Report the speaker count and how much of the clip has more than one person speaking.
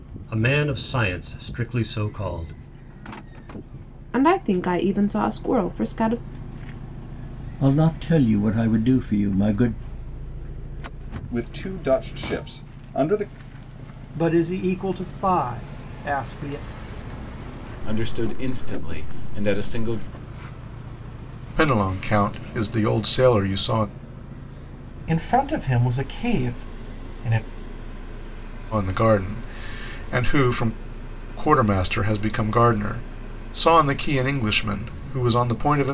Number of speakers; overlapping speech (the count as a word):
eight, no overlap